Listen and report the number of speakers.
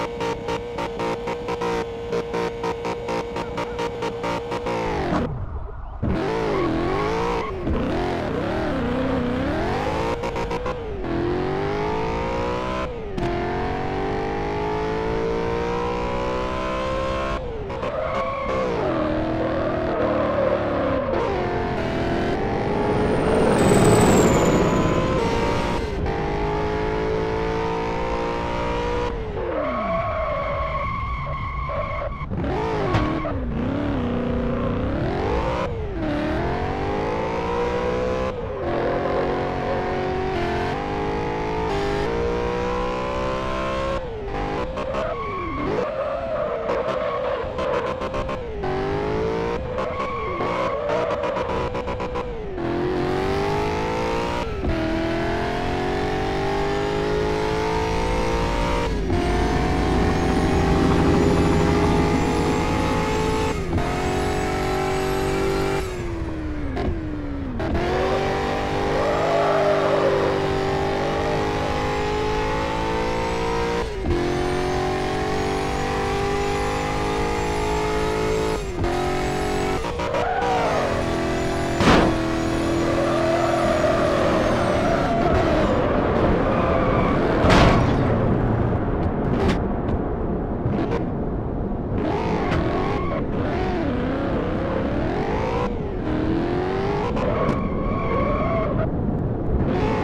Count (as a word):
zero